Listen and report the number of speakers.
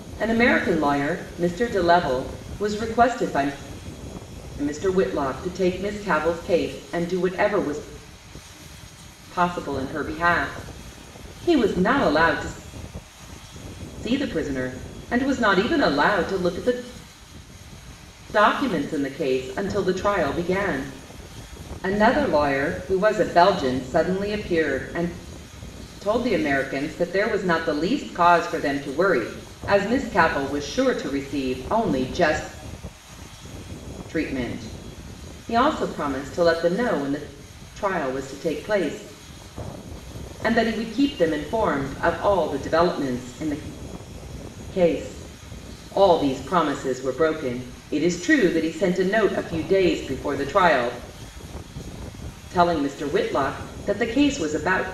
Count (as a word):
one